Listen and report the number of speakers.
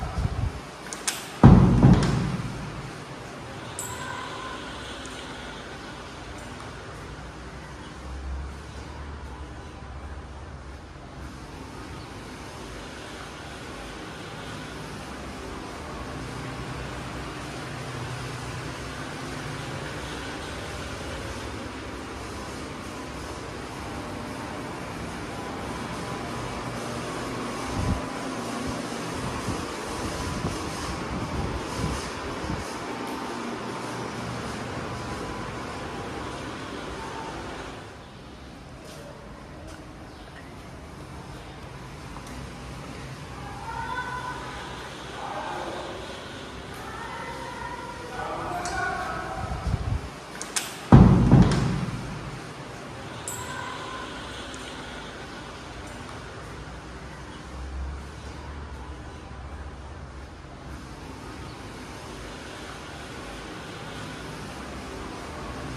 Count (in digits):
0